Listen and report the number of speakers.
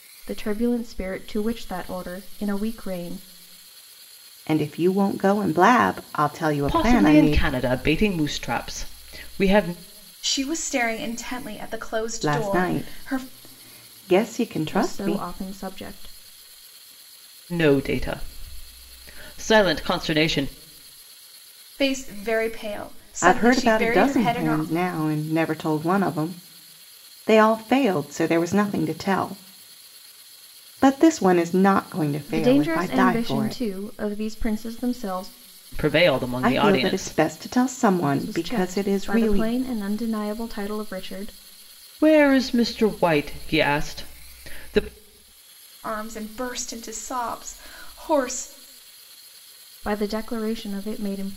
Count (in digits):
4